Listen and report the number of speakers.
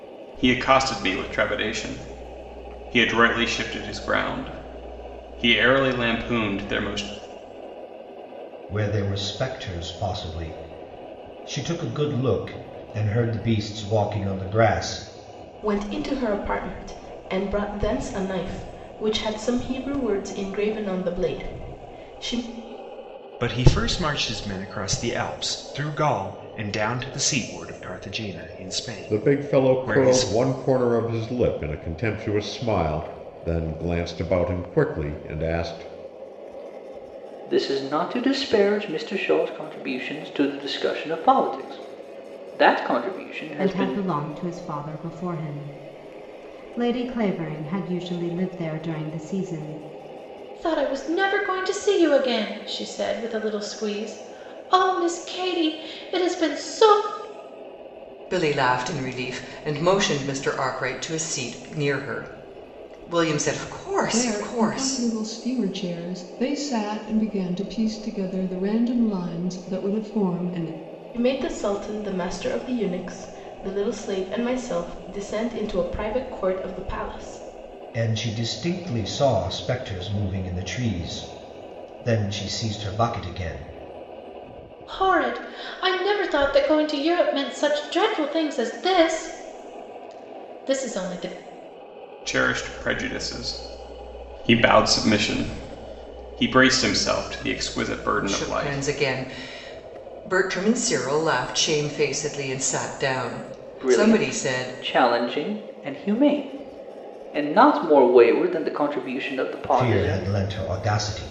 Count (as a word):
ten